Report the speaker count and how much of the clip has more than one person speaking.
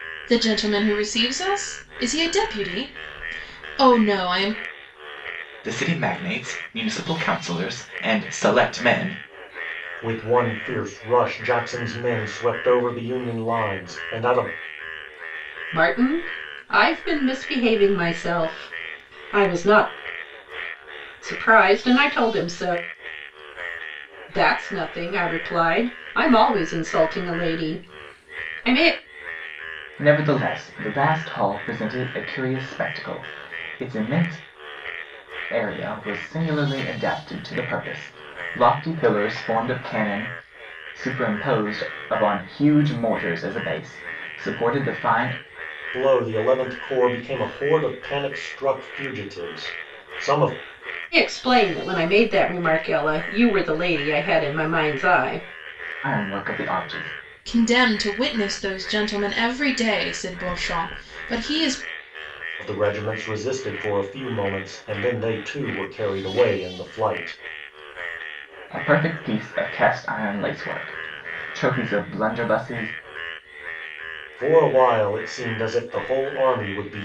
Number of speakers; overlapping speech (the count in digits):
4, no overlap